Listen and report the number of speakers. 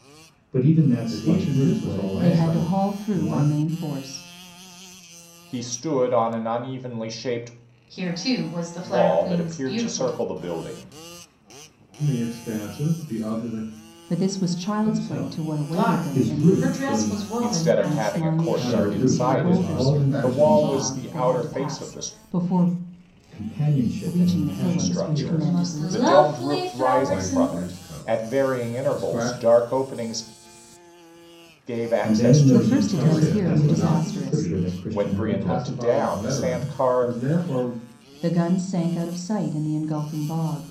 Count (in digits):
5